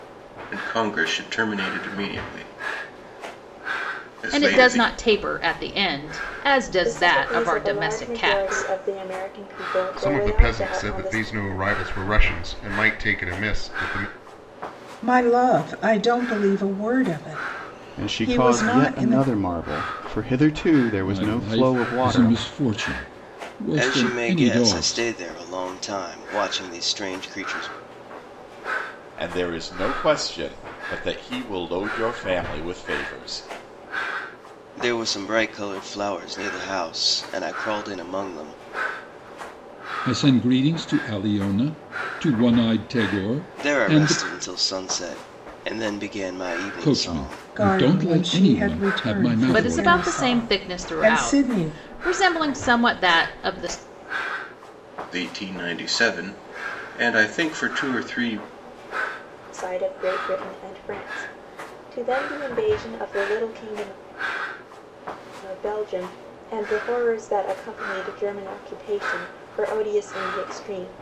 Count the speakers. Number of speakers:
9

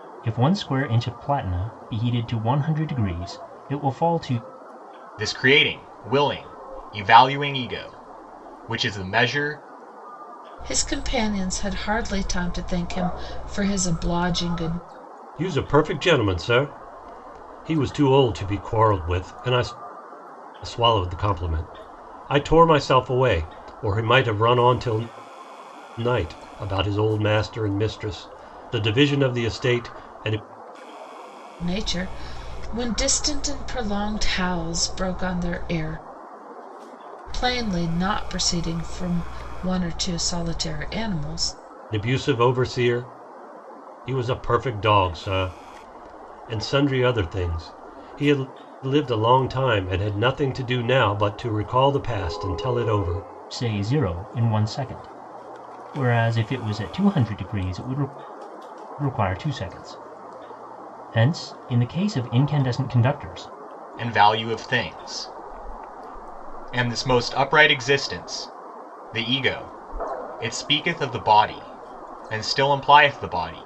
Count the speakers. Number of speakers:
4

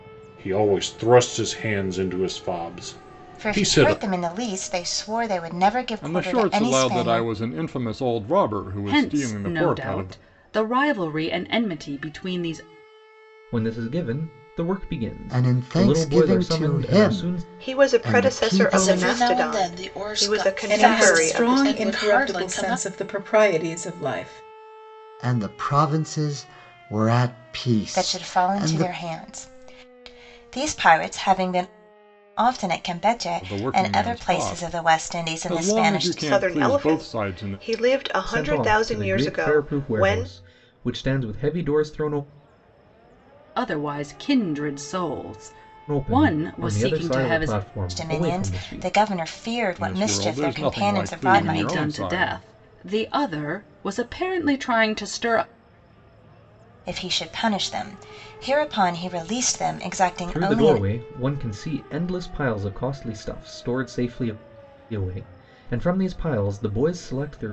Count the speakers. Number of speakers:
9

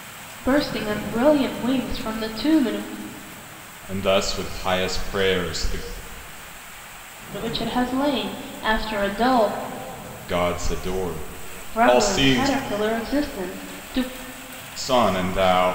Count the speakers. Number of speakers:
2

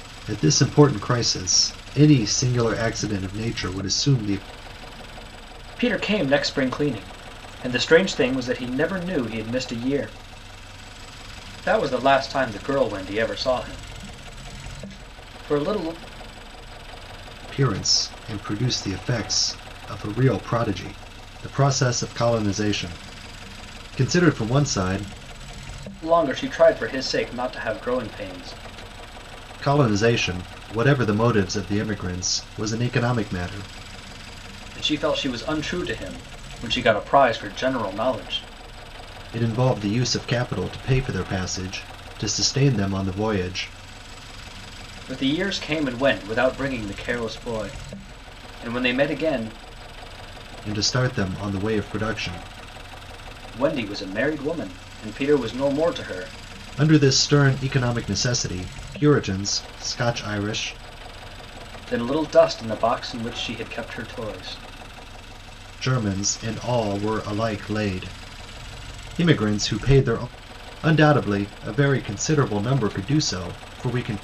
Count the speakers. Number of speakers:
2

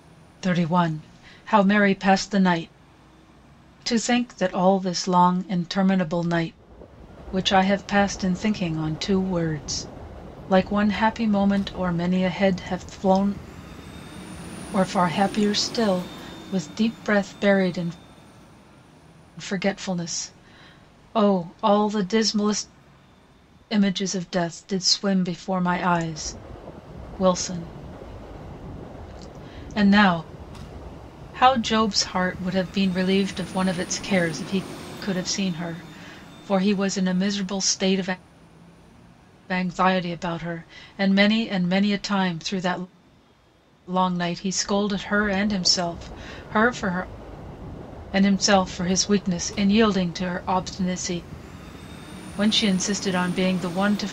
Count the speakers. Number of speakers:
1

